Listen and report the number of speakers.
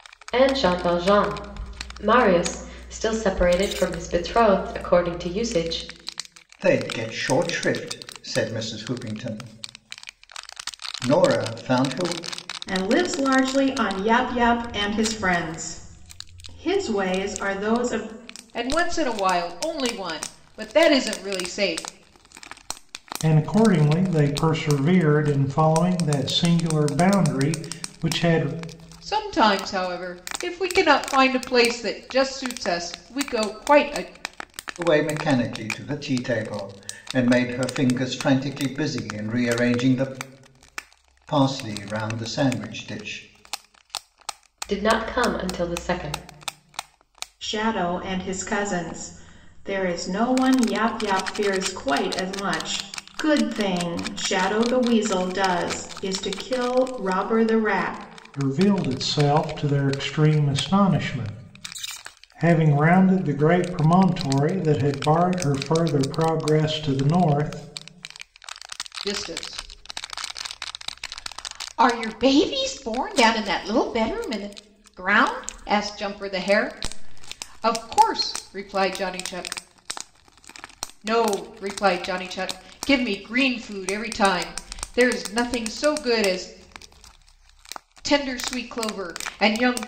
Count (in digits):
5